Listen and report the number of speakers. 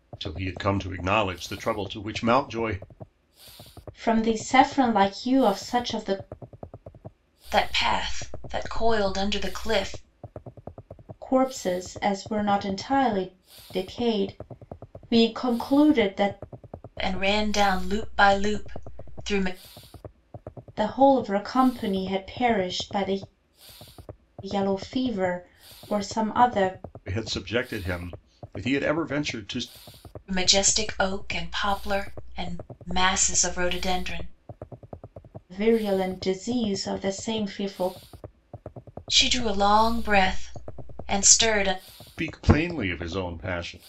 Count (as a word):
three